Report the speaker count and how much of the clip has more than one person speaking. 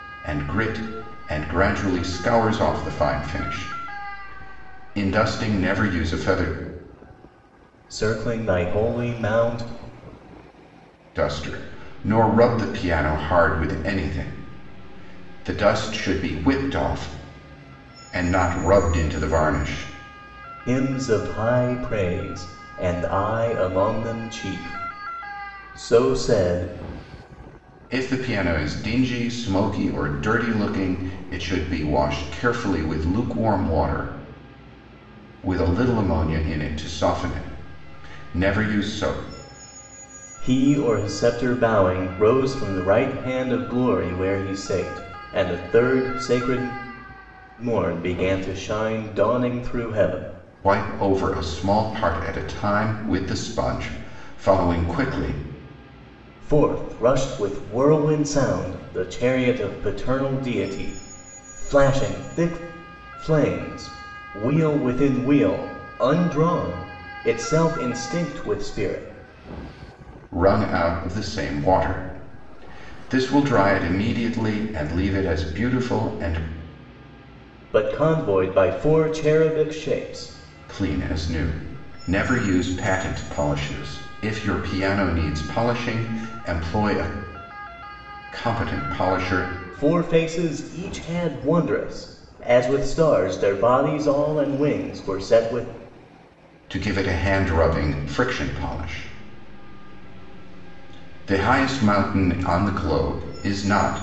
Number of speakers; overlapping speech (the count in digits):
2, no overlap